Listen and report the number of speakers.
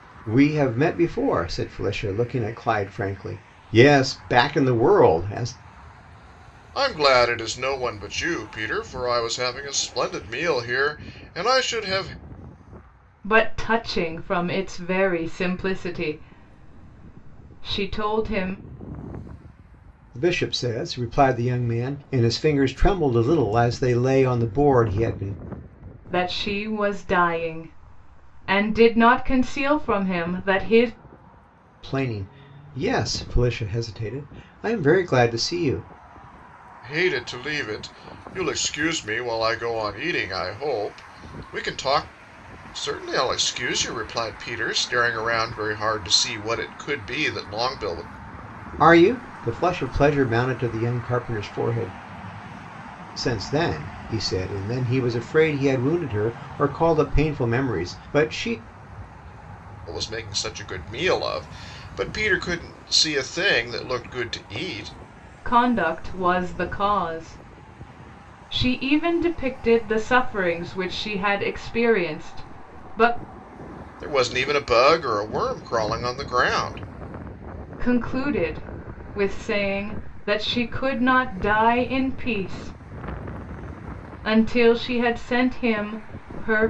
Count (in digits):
3